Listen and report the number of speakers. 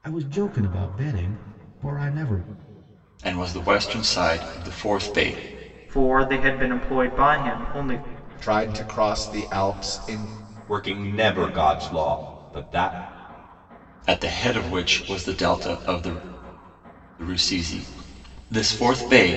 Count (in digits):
5